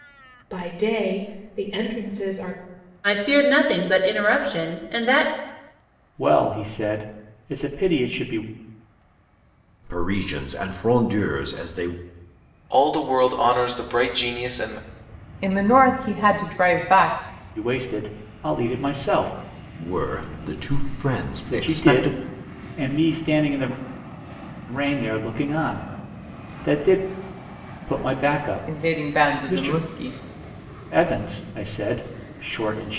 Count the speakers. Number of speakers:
6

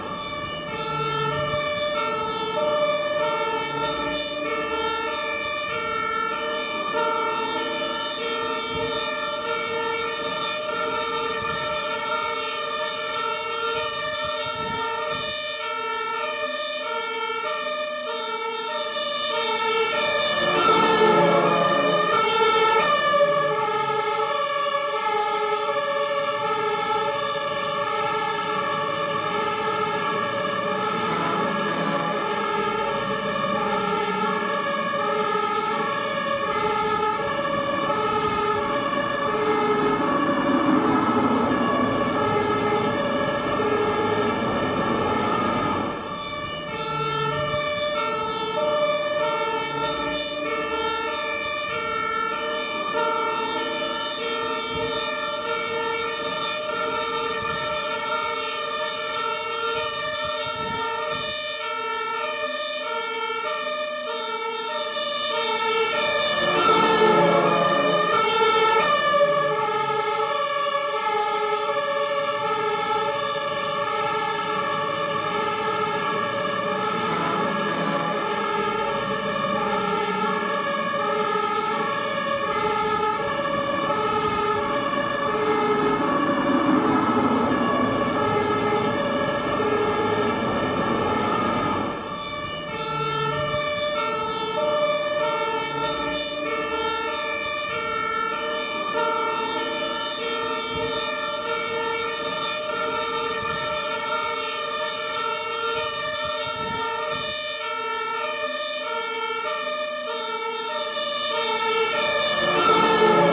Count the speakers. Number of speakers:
0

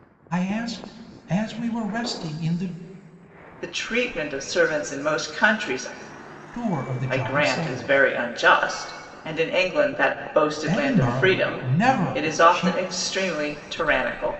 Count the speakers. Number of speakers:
2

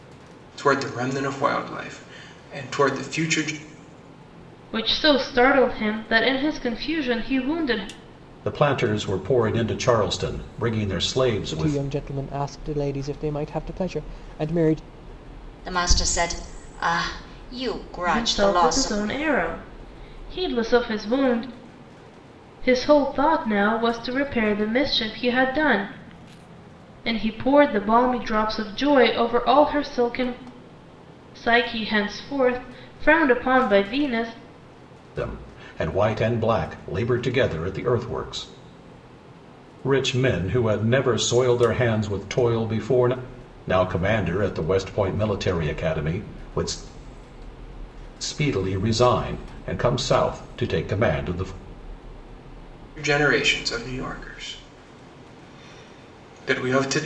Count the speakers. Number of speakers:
5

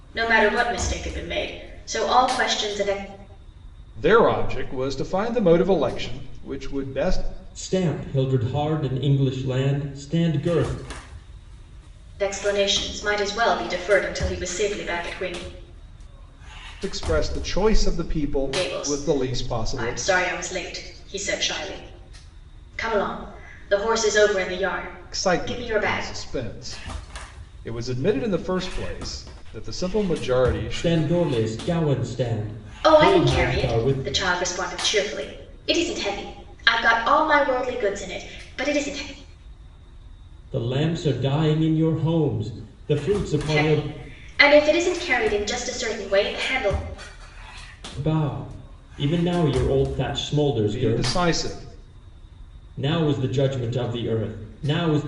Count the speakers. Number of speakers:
3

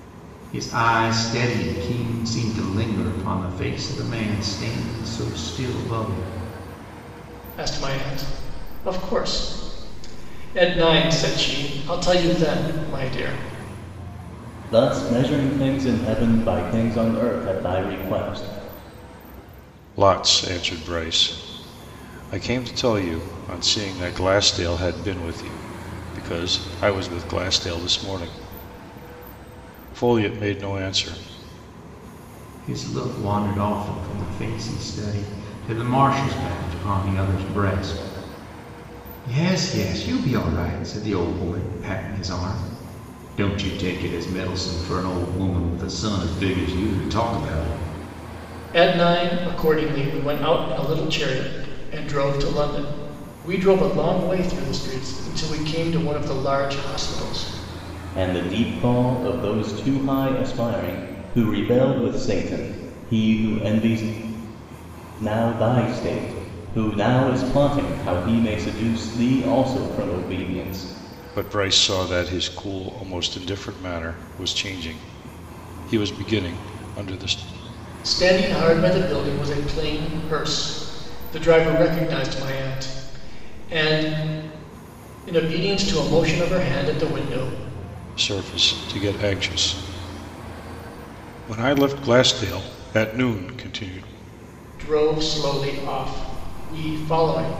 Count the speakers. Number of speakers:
4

